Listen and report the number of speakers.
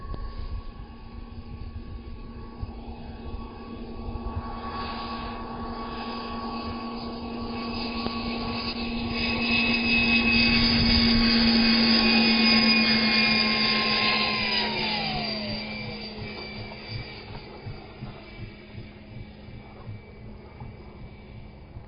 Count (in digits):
0